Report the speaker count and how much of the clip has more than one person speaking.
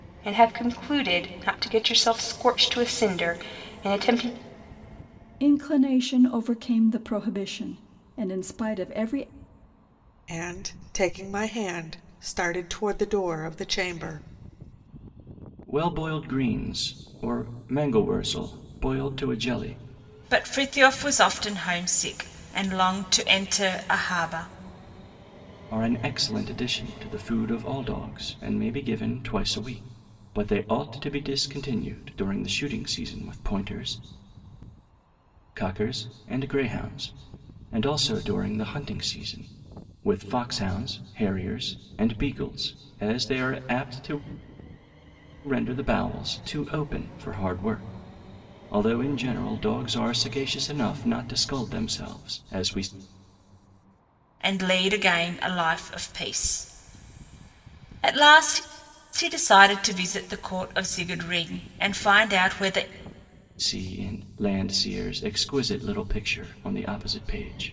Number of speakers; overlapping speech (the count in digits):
5, no overlap